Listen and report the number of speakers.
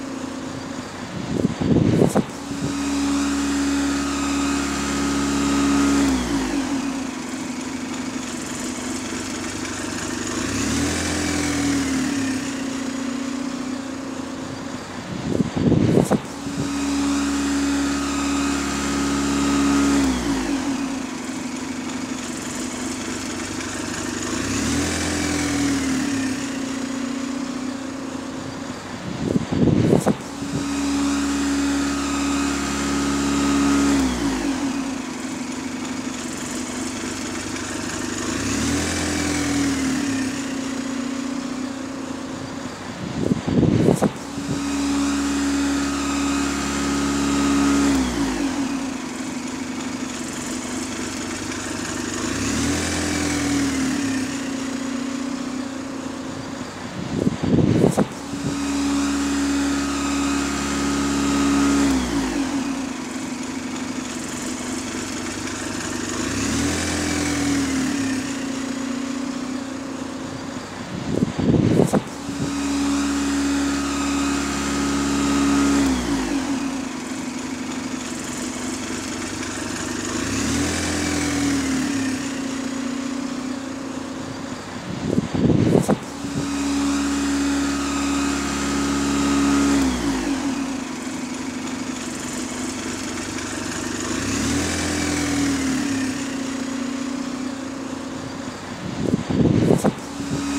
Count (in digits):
0